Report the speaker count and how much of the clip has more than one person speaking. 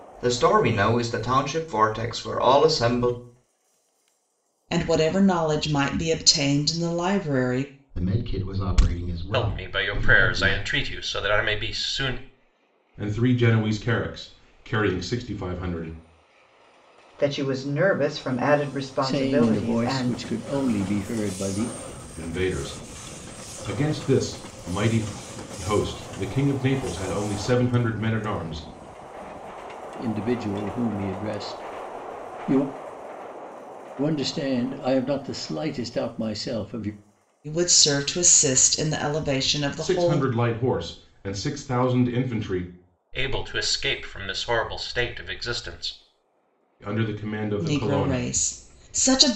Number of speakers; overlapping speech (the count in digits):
7, about 7%